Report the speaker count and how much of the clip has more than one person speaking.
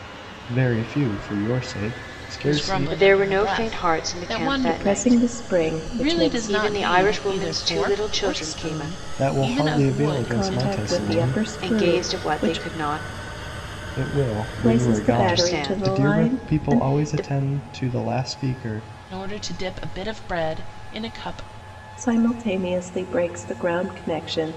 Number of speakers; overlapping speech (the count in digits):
4, about 50%